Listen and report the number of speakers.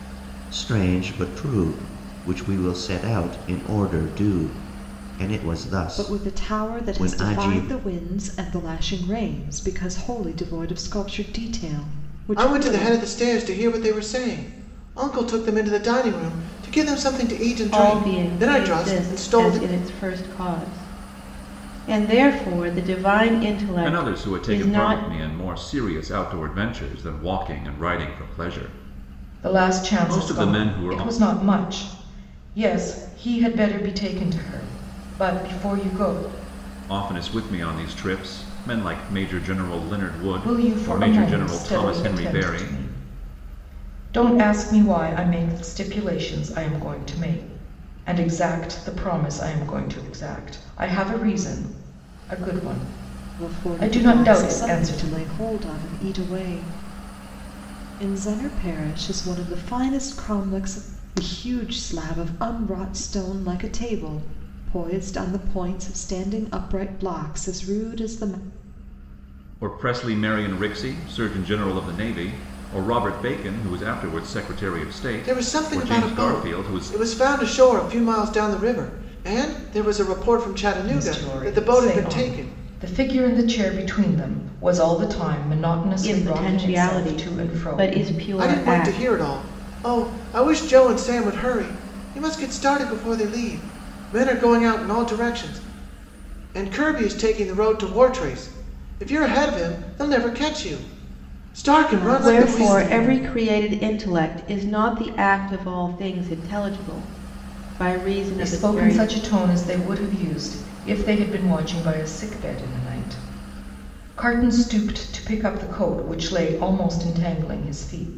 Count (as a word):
six